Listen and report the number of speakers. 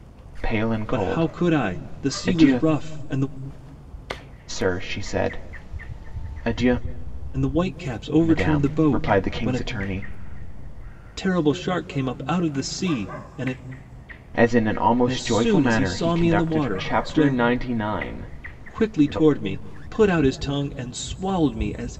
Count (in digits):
2